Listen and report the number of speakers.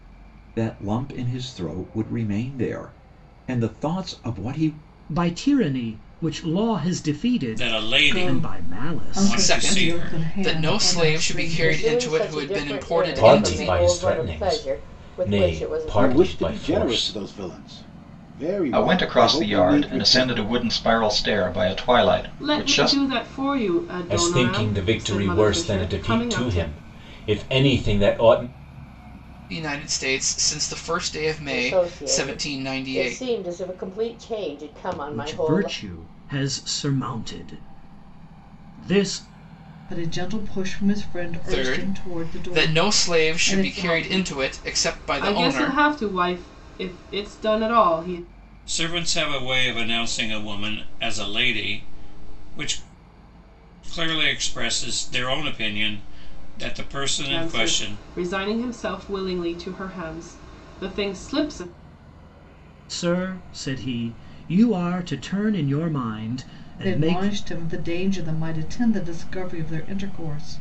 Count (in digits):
10